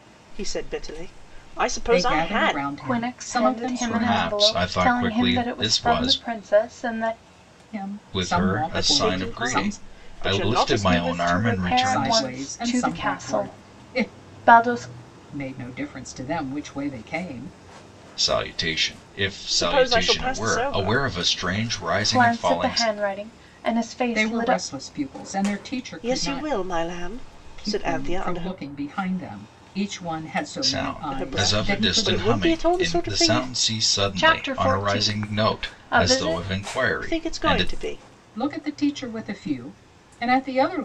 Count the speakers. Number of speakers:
four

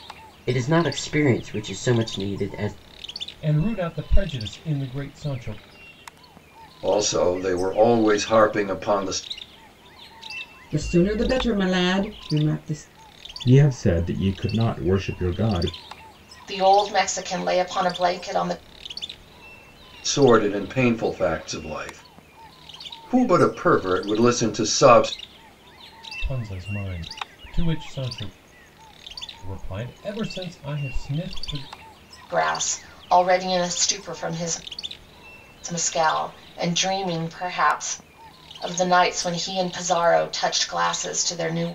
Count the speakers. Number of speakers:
six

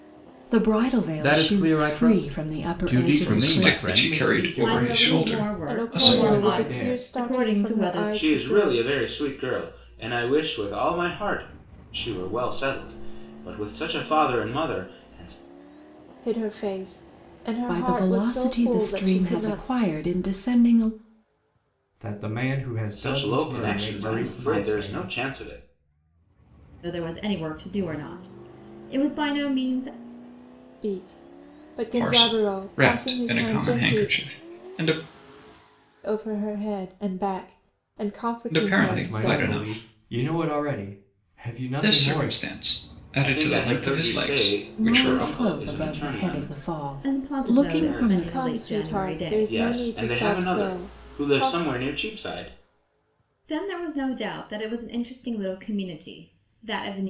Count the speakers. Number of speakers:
seven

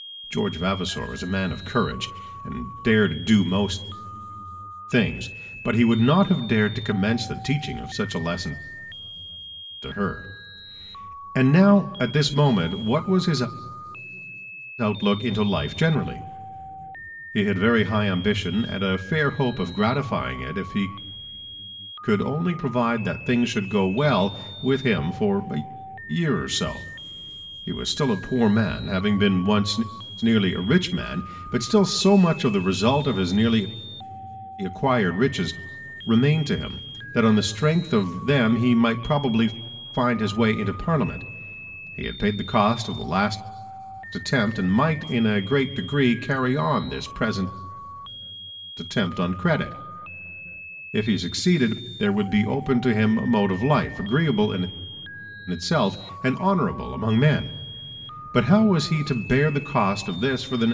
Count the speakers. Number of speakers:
one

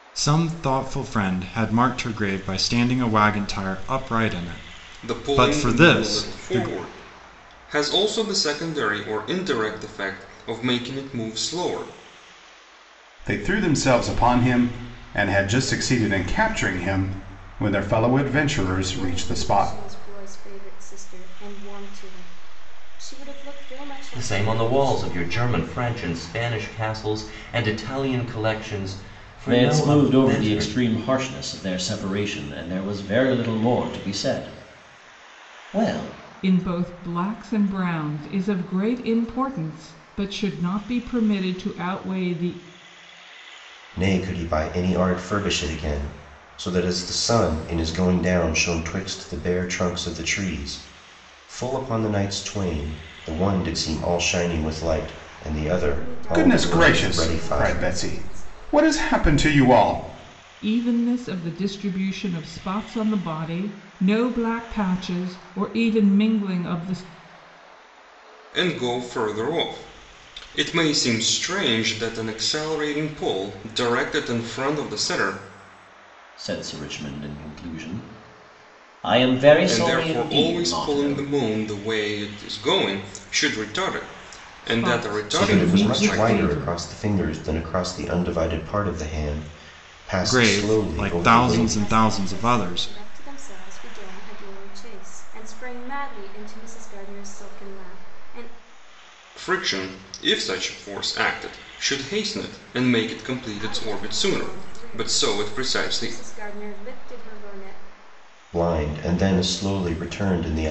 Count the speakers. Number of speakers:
eight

